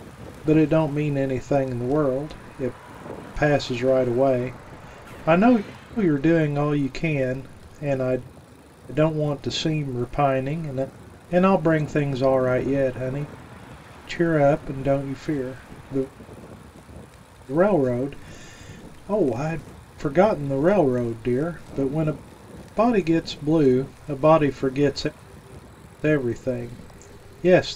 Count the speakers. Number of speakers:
one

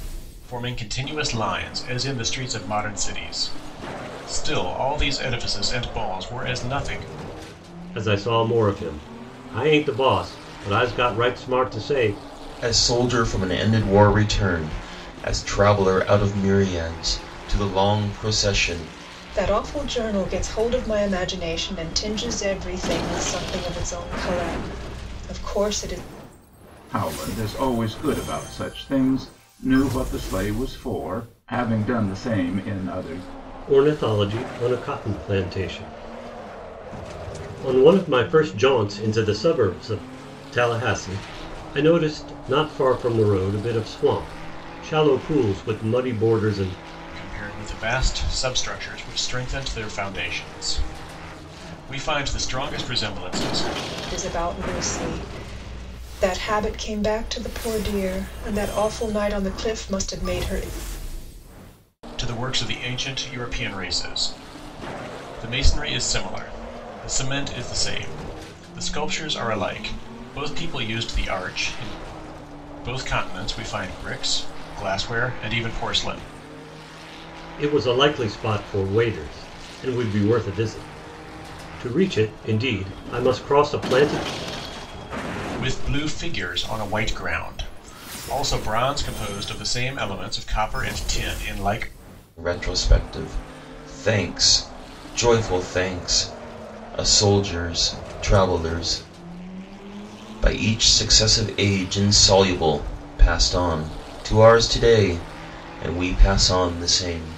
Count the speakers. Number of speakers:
five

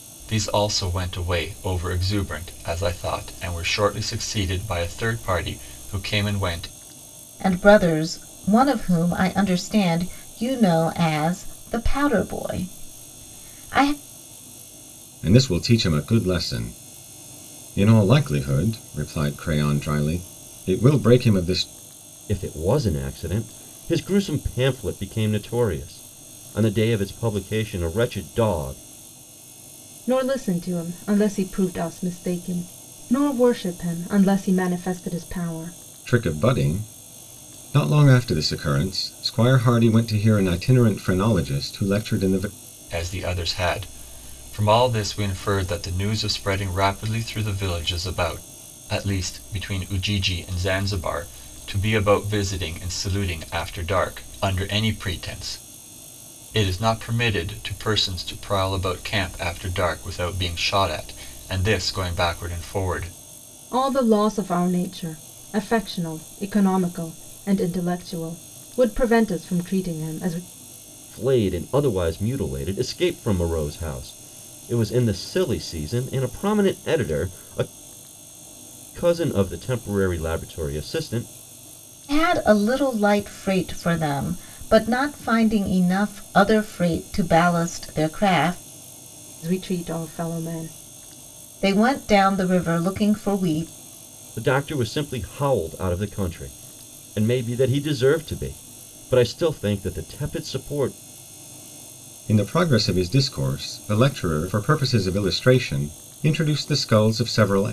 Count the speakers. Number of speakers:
five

